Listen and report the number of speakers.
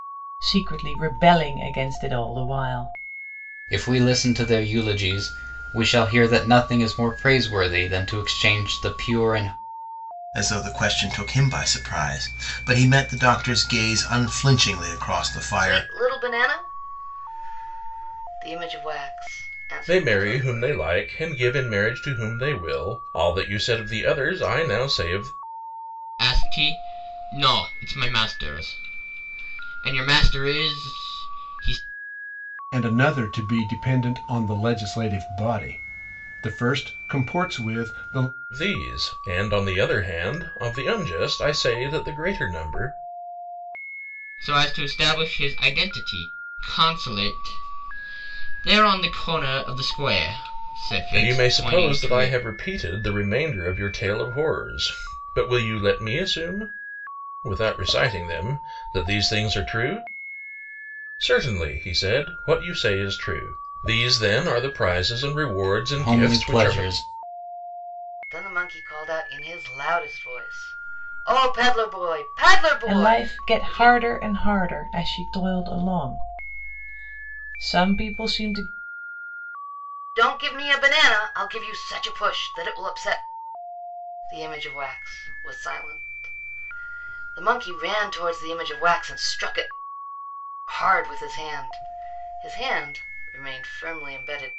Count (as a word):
seven